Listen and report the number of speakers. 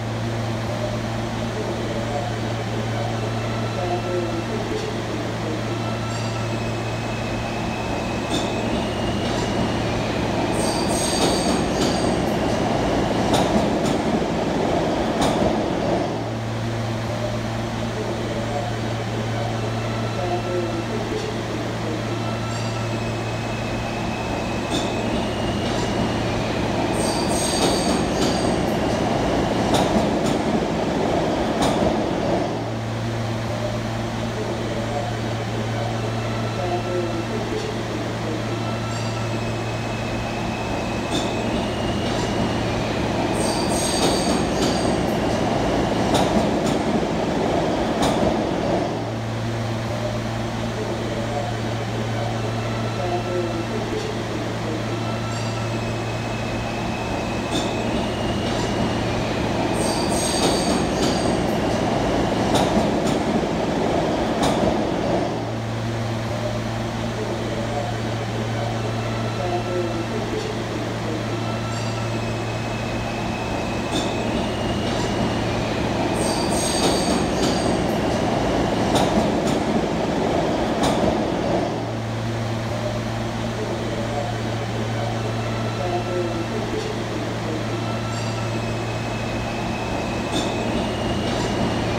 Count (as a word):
zero